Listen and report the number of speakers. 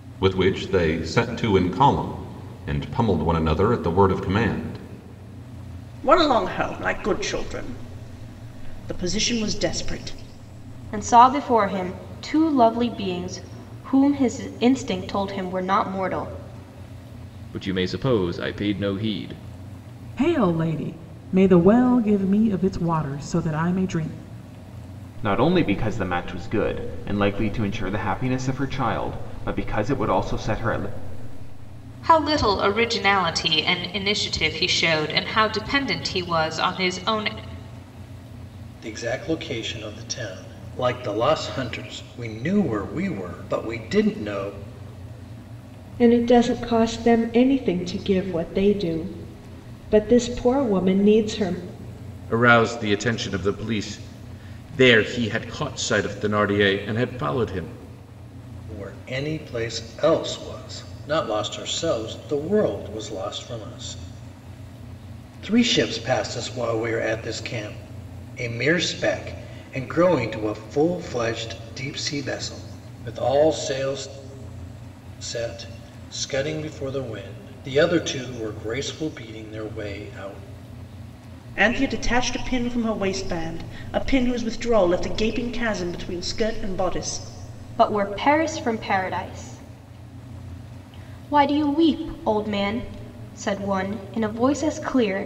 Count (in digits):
10